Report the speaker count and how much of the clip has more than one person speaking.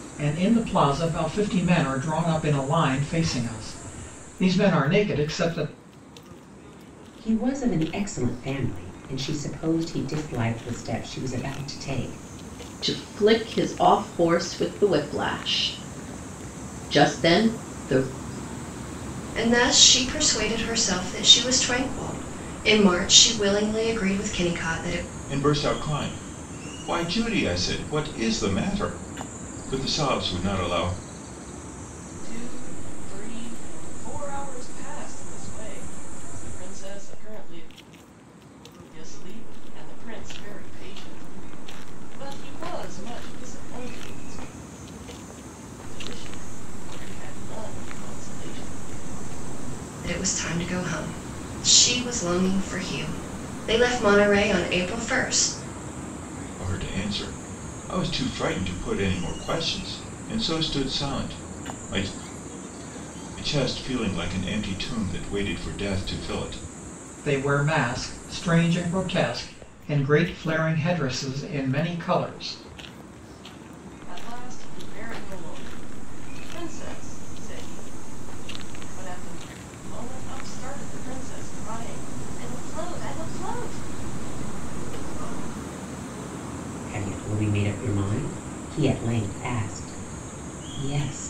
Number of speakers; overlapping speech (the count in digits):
6, no overlap